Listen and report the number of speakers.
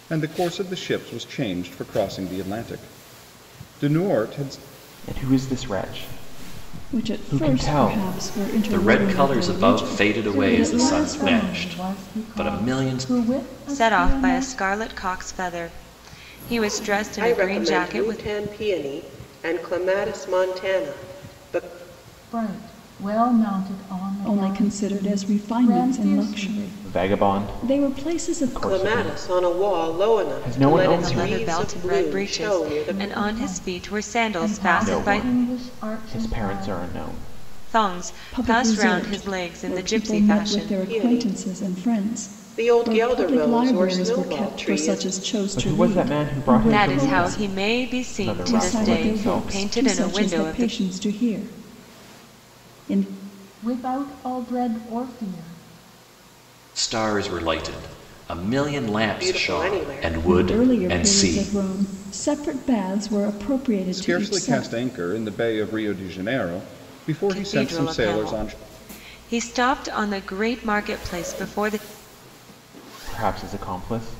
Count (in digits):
7